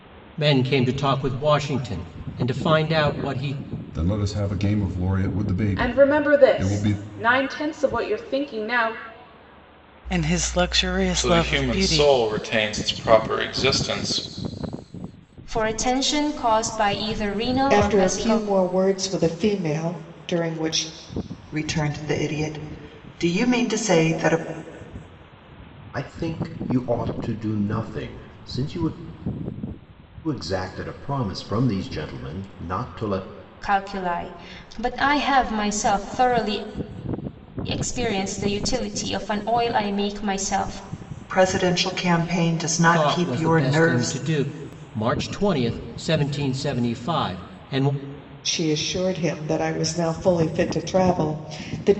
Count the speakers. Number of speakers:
9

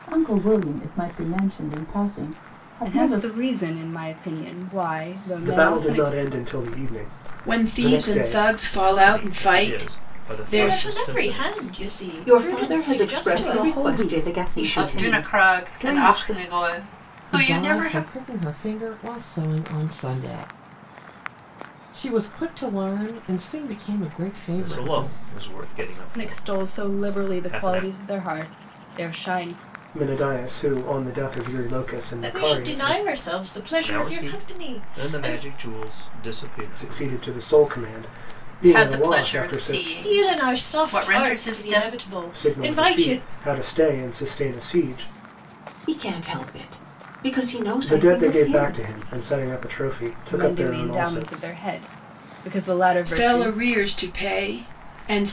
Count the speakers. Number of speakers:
10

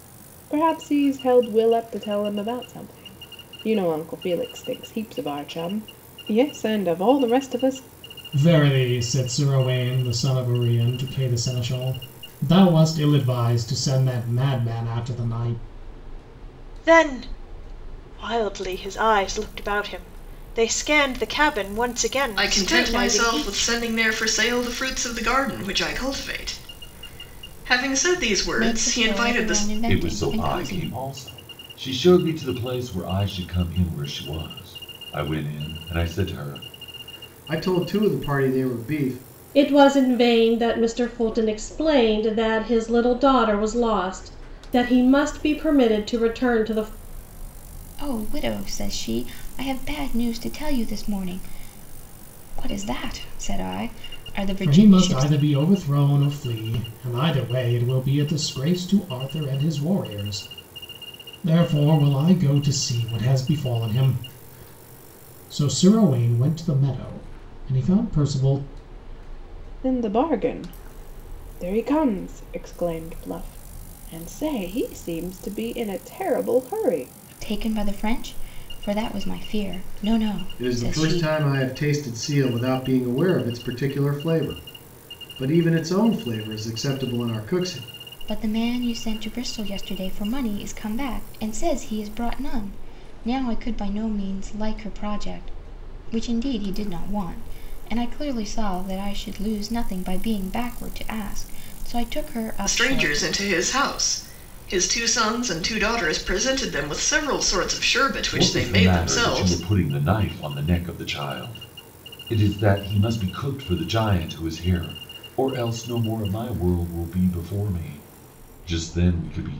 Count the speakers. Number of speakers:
8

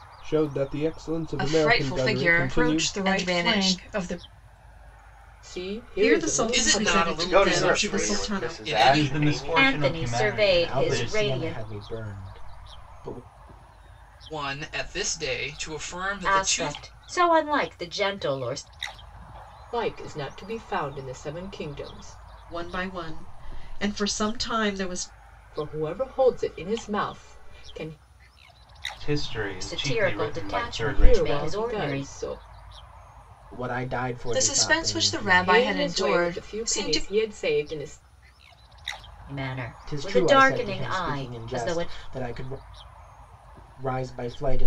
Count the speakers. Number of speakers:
10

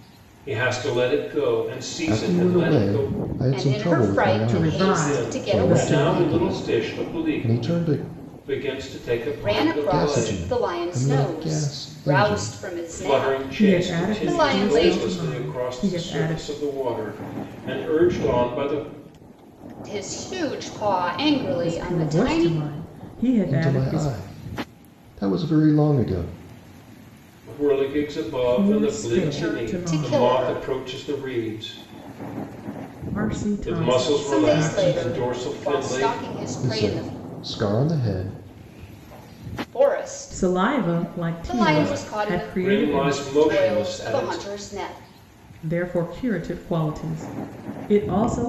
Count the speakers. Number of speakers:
4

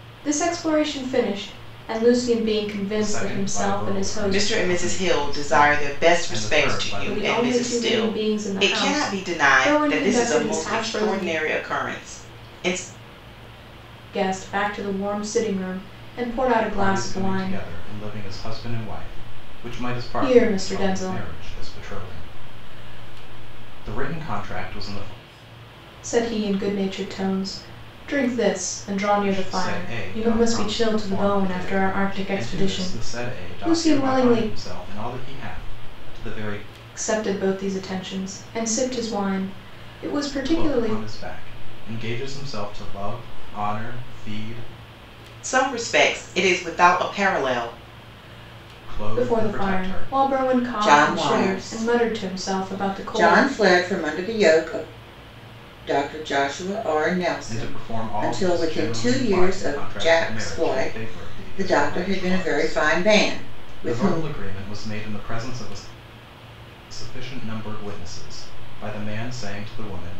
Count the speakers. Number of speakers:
3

